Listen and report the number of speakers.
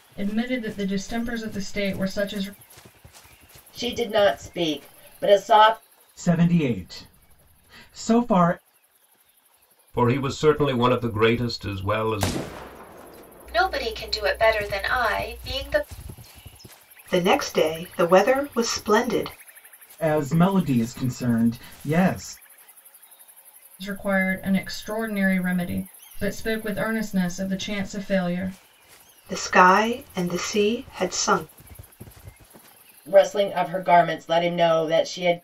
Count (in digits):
6